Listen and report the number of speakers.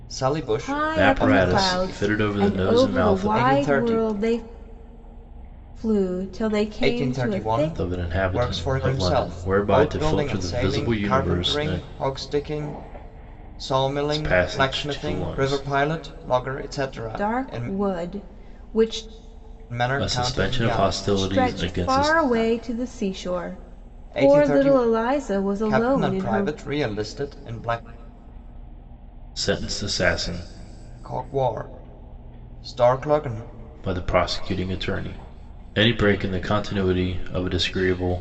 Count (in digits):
3